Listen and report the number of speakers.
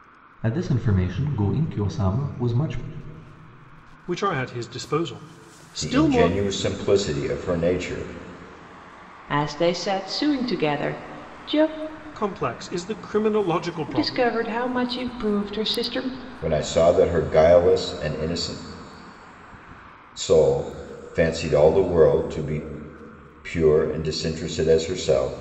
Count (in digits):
4